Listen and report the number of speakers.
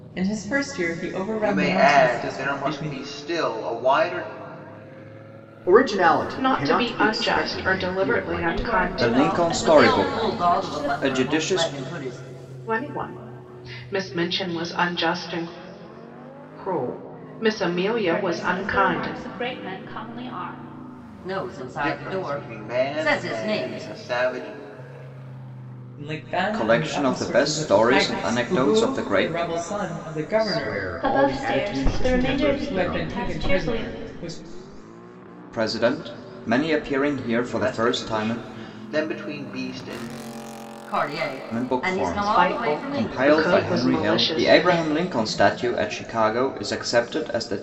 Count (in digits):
7